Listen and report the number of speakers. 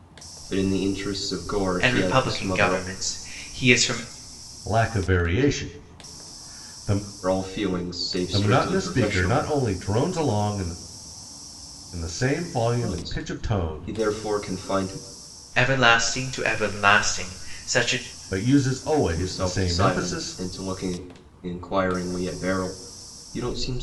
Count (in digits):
3